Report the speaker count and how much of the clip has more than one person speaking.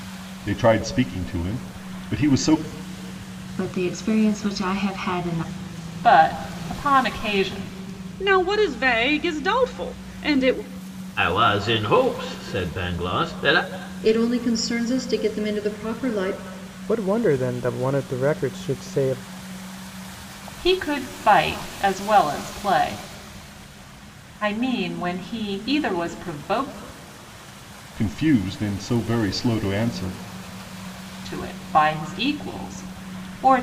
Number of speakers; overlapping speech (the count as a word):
seven, no overlap